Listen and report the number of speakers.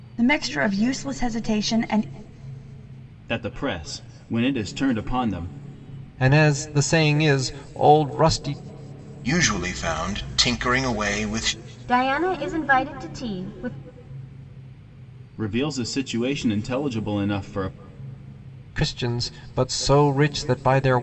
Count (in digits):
5